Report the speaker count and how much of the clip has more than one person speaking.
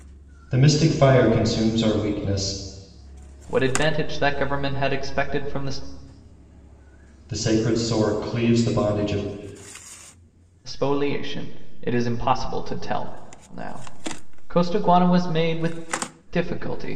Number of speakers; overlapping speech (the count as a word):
two, no overlap